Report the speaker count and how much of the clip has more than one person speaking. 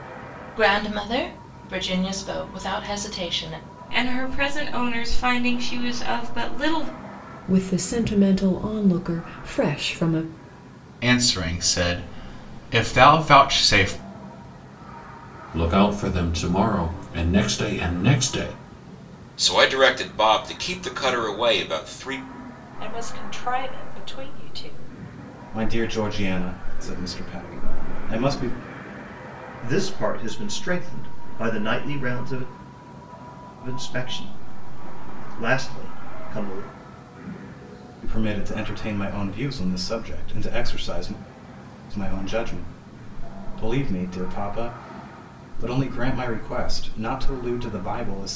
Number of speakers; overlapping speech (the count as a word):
nine, no overlap